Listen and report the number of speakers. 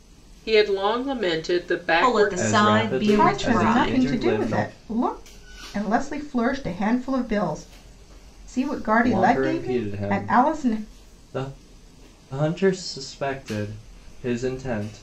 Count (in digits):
4